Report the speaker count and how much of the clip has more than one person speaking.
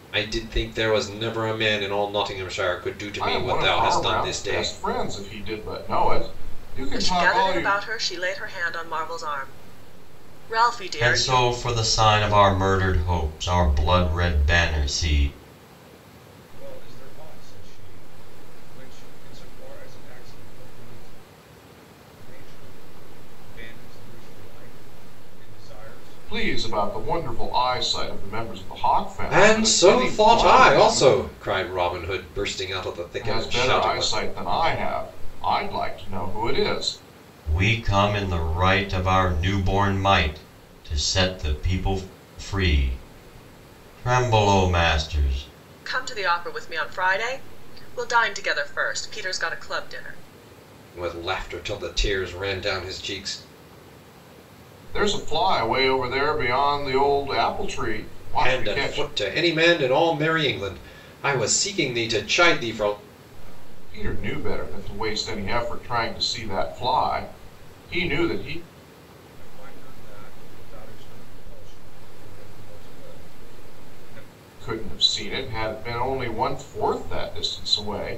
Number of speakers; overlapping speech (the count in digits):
5, about 11%